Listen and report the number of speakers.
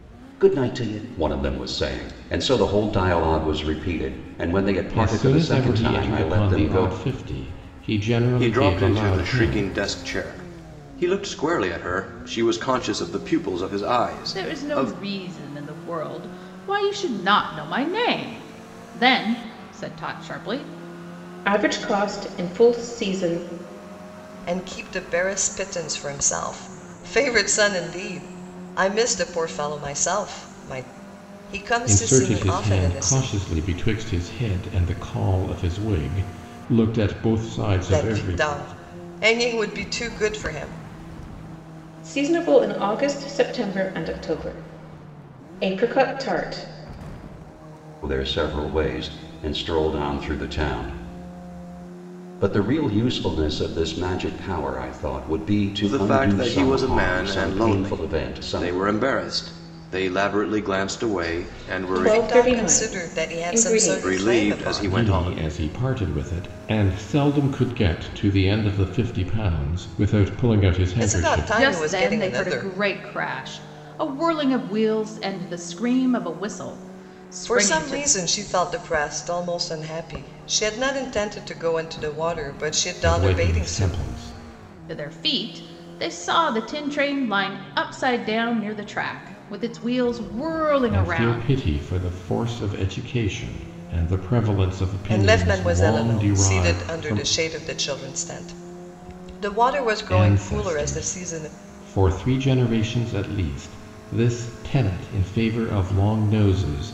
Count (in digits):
6